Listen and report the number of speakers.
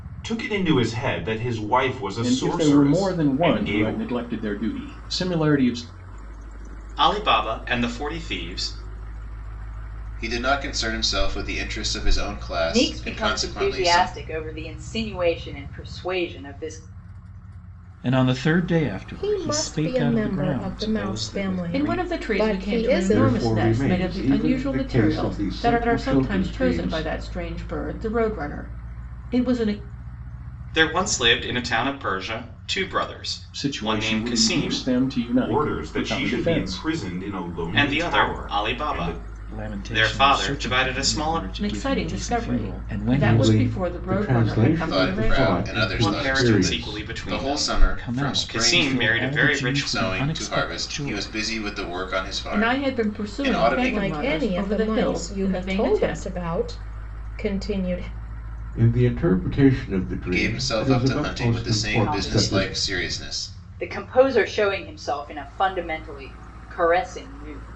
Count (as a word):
nine